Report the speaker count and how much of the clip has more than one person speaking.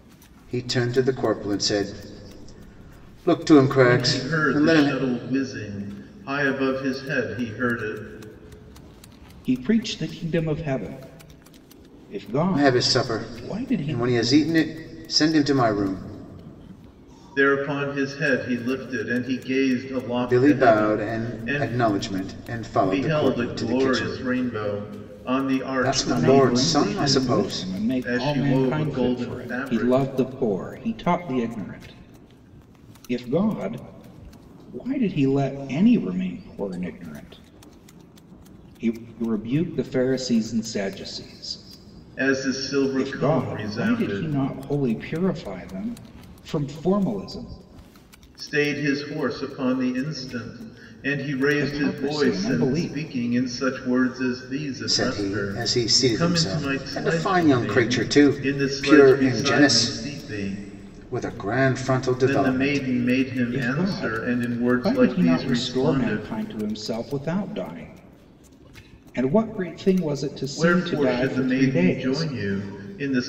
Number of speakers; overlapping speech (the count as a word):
three, about 33%